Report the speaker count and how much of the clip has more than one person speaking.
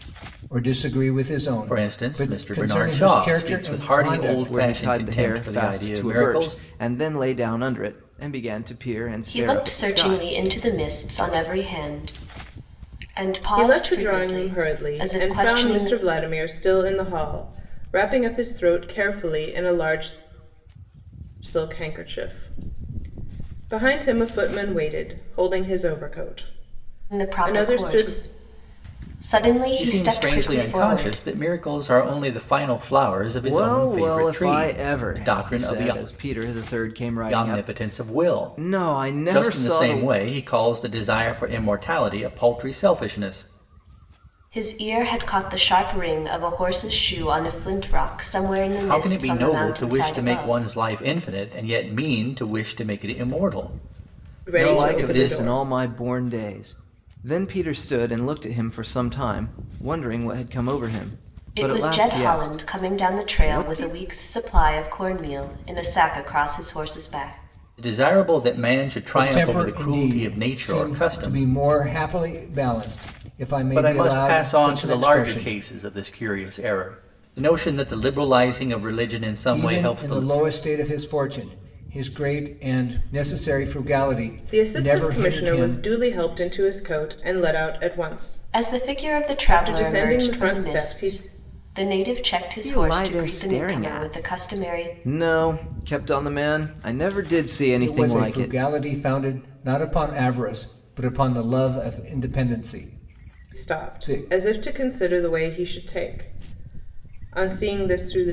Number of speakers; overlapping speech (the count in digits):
5, about 32%